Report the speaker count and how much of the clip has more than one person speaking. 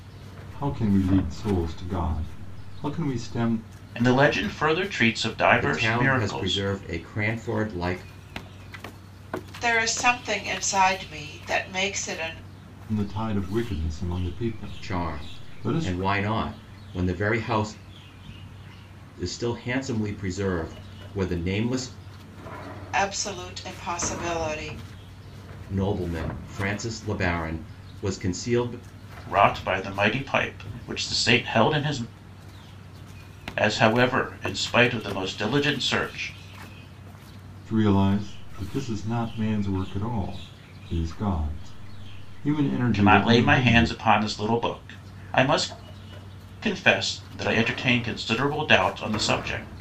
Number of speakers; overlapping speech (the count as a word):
four, about 7%